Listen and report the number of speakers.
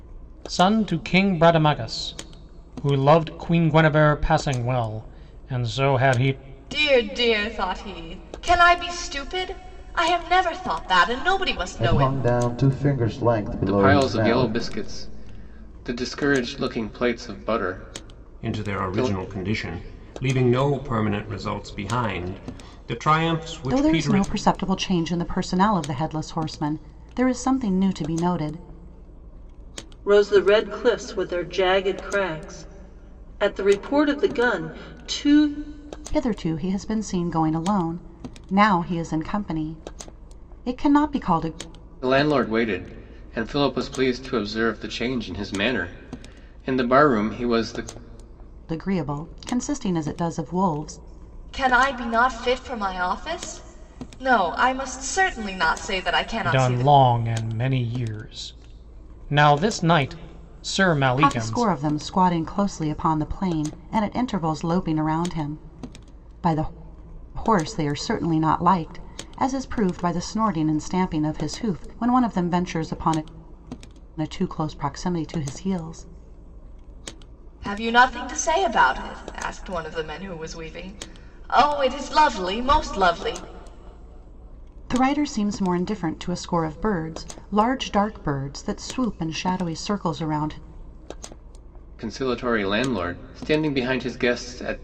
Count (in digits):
7